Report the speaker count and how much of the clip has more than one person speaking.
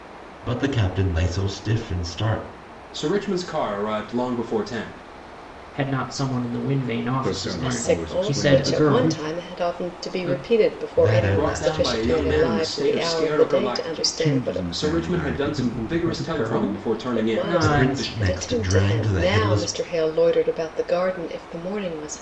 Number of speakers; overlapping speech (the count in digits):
5, about 54%